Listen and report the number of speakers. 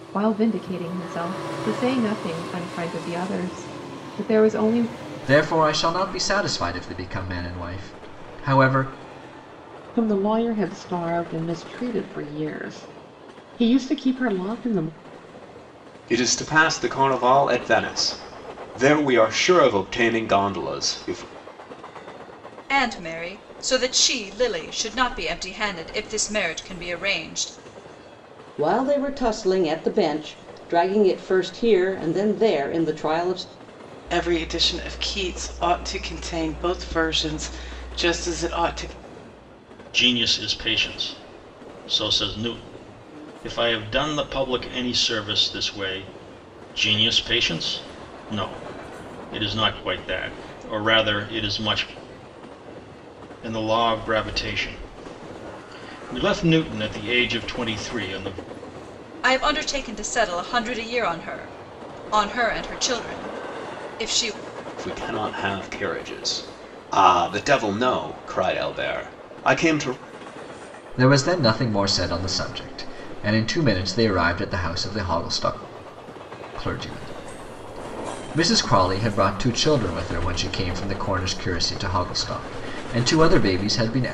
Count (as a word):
eight